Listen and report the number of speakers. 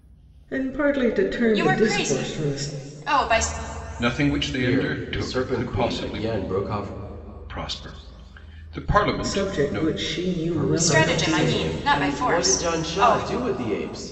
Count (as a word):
four